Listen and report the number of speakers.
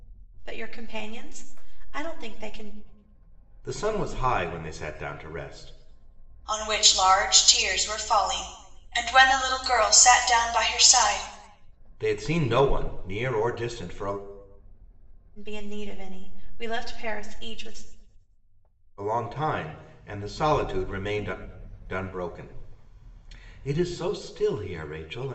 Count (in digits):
3